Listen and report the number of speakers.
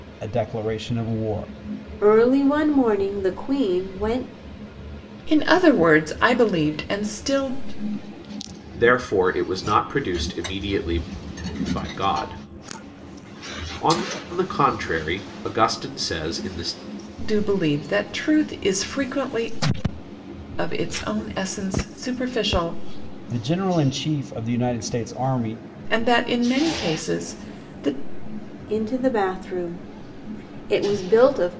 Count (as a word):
four